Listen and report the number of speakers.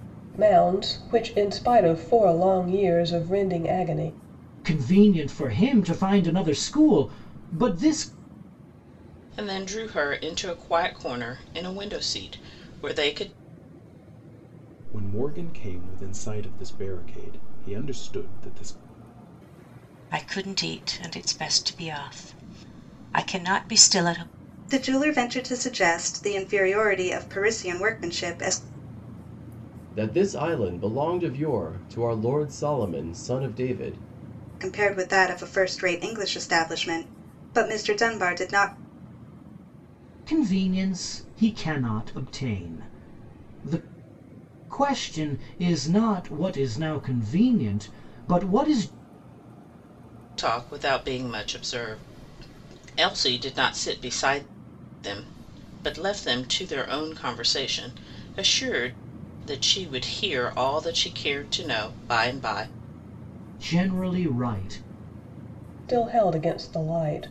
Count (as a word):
seven